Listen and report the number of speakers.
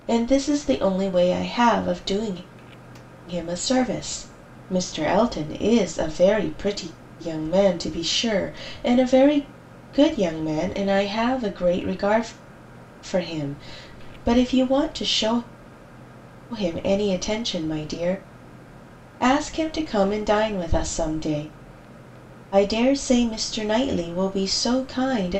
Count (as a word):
one